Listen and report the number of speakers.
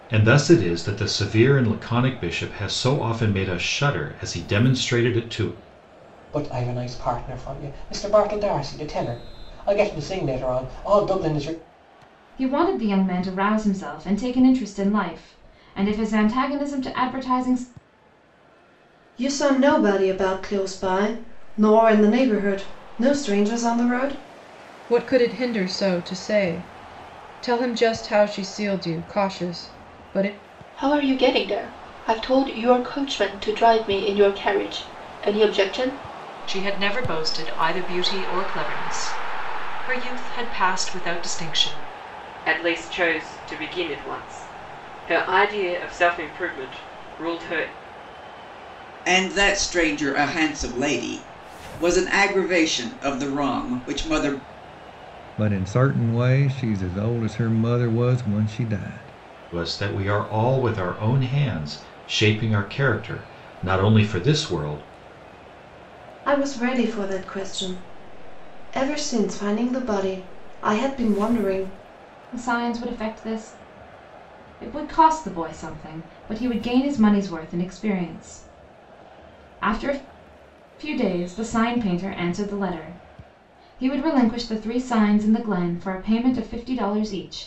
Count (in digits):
10